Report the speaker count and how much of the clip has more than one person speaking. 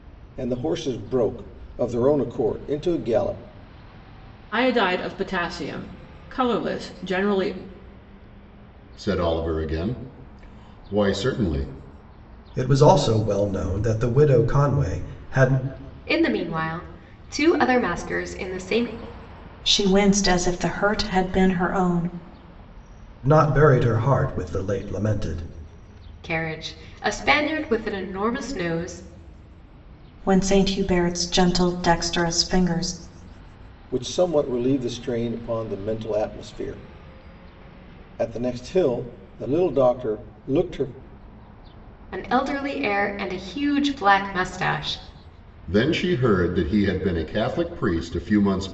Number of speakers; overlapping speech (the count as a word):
six, no overlap